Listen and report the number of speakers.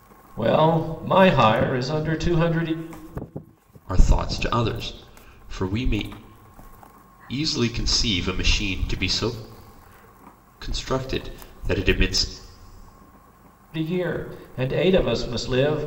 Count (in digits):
2